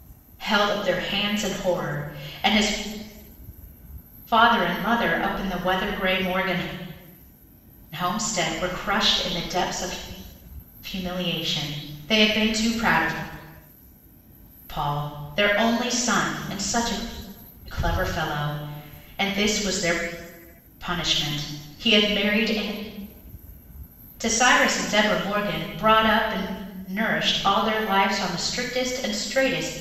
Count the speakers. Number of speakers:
1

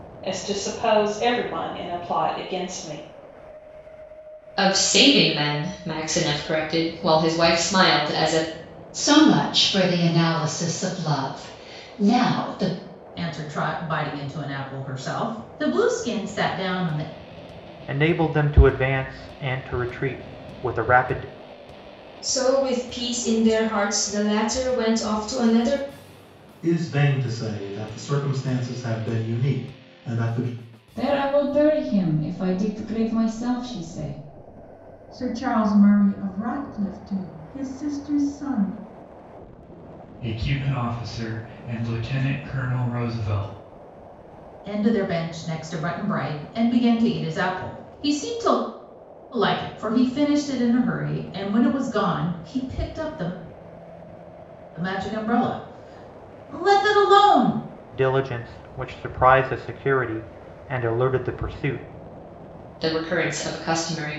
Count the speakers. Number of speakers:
10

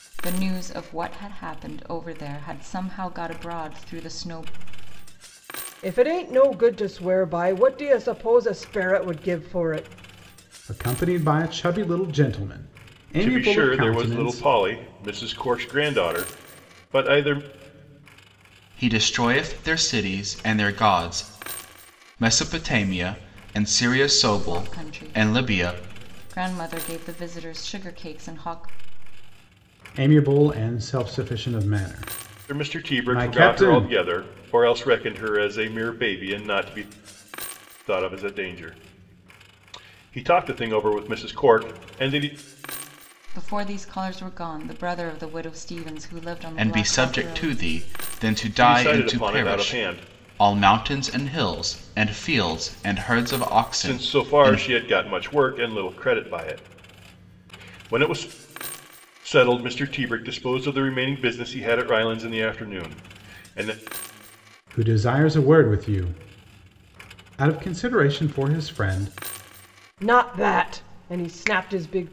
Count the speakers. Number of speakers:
5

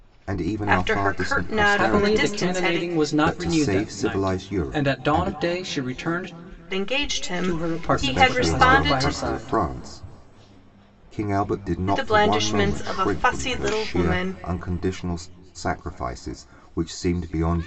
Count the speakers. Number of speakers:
3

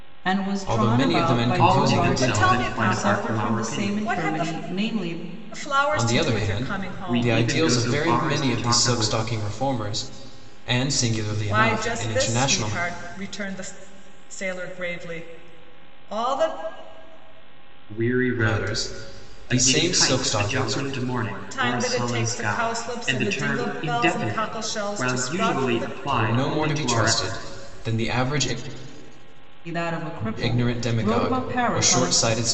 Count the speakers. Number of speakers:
4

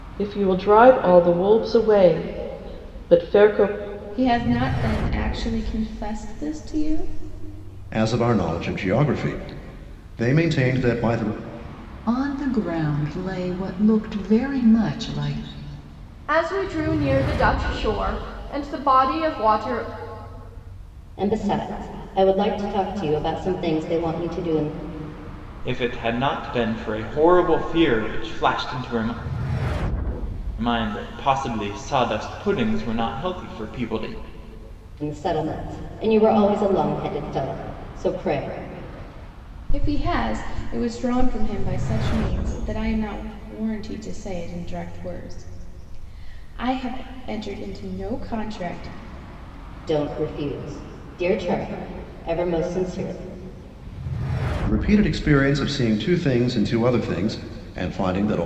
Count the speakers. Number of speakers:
7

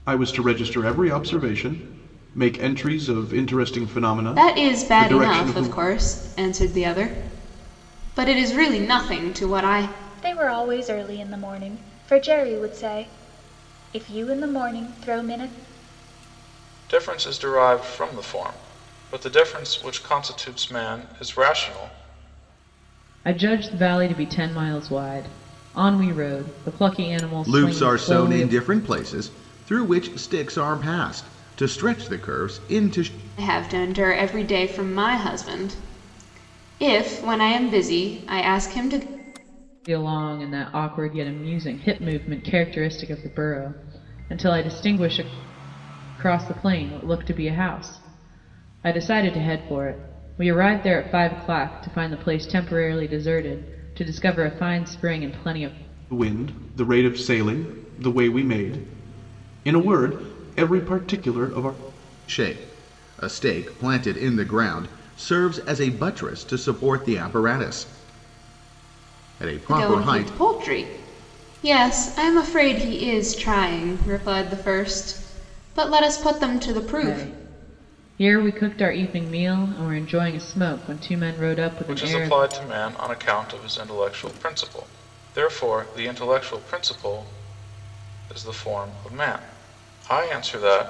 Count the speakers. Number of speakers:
6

